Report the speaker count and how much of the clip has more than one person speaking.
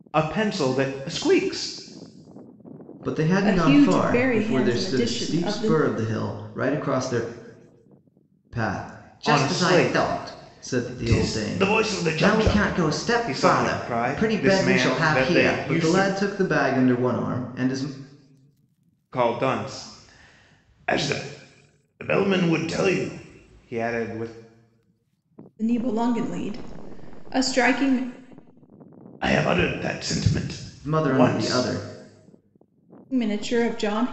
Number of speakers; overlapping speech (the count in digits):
3, about 29%